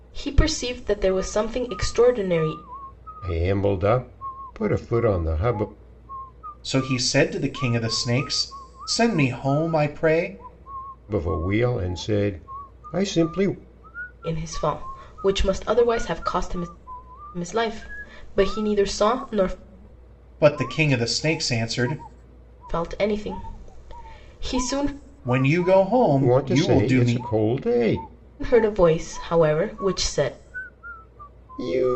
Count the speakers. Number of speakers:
three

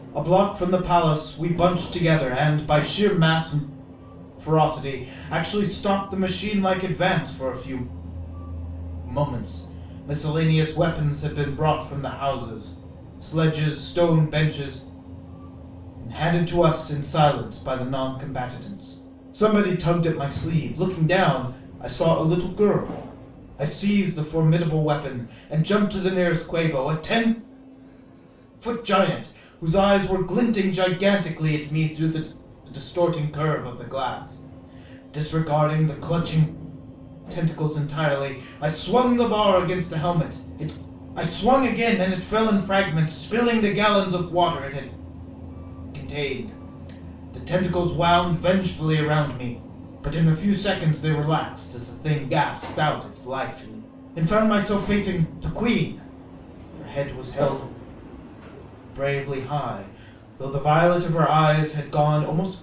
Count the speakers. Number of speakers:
one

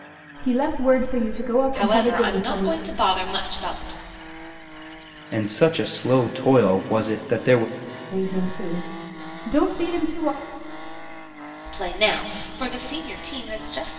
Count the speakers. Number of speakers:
three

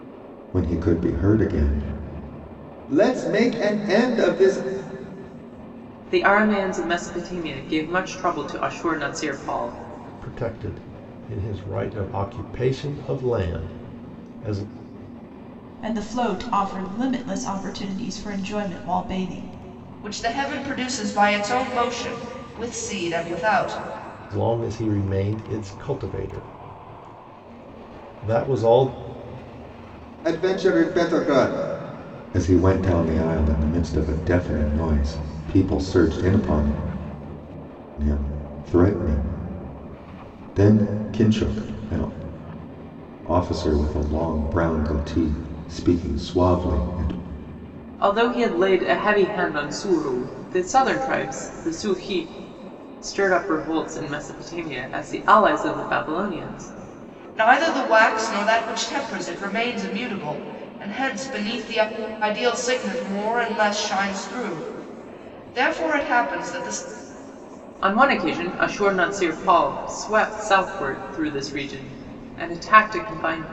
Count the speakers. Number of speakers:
five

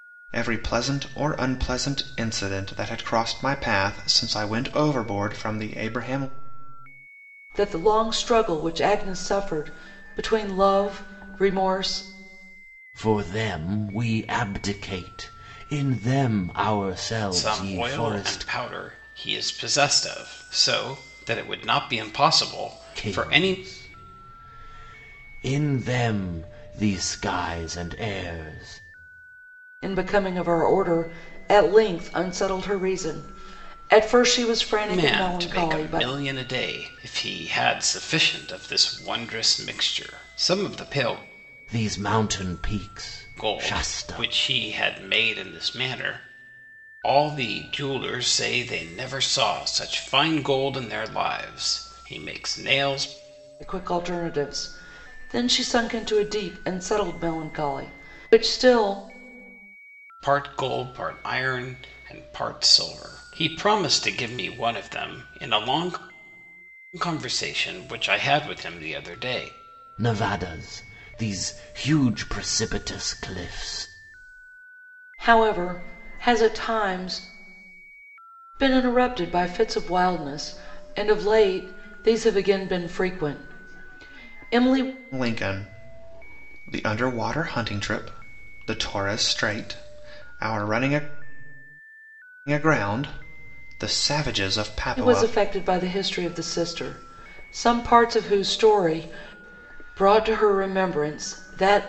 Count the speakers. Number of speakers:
four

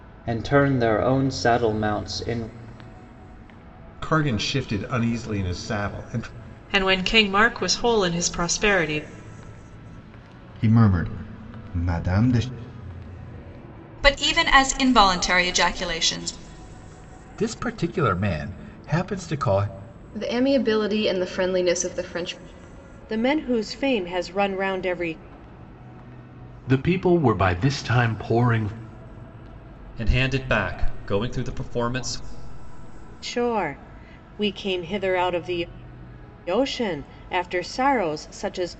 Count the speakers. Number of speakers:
ten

